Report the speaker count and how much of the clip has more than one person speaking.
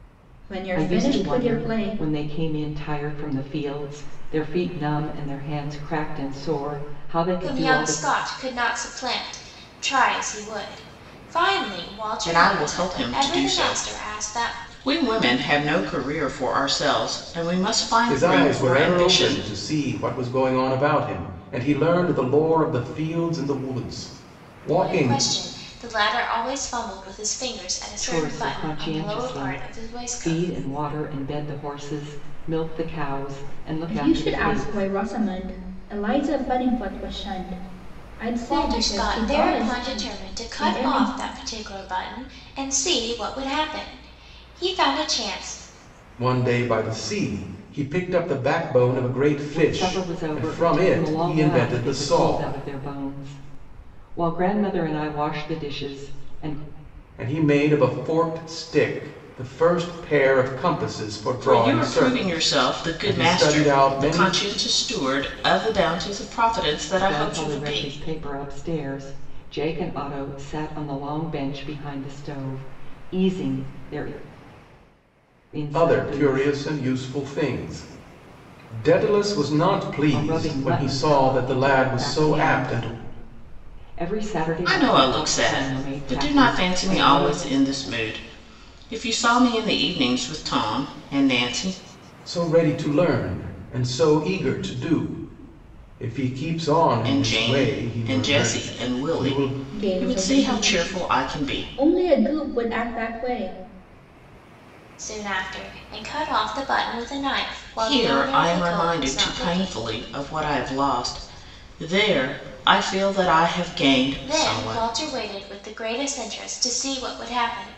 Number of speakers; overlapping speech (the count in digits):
5, about 28%